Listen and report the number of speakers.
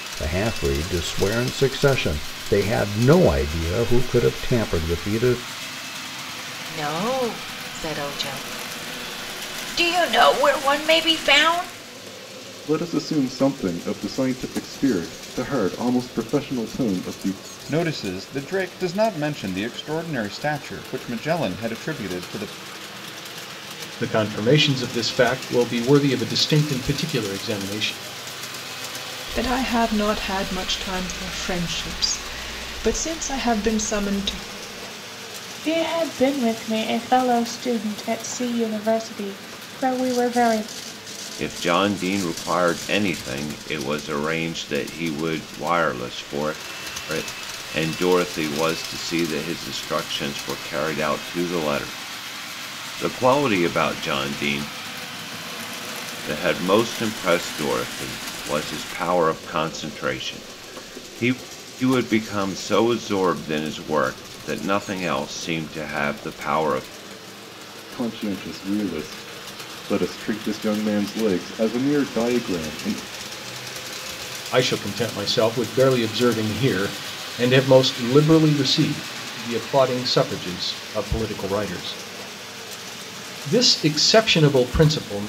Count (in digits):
8